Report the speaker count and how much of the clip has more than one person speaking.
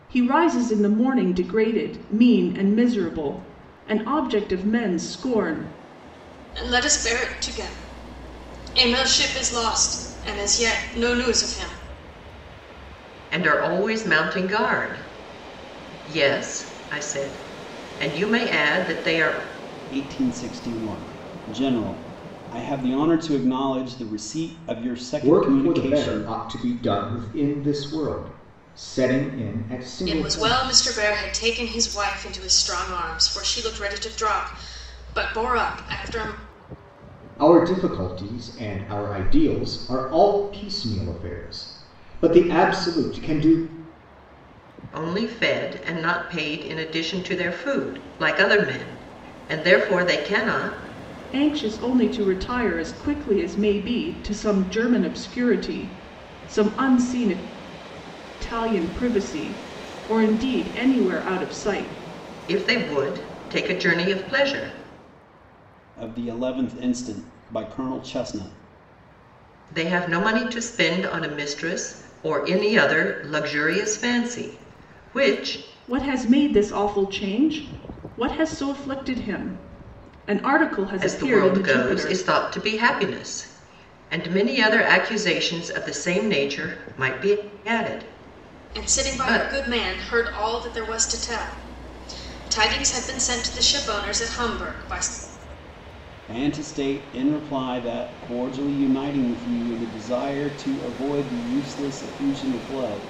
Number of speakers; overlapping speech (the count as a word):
five, about 4%